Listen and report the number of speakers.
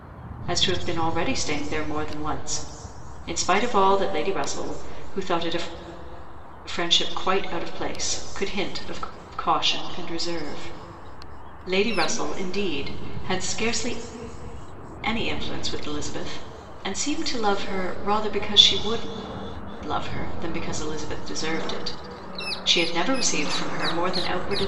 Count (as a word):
one